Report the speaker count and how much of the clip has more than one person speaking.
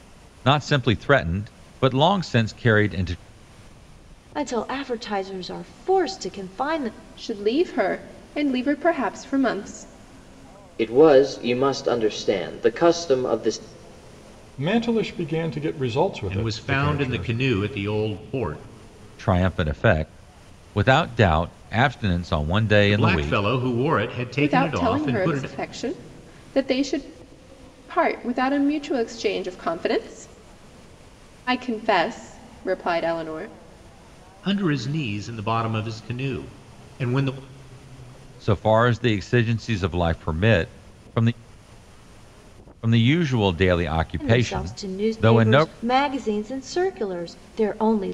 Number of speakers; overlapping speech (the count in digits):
6, about 9%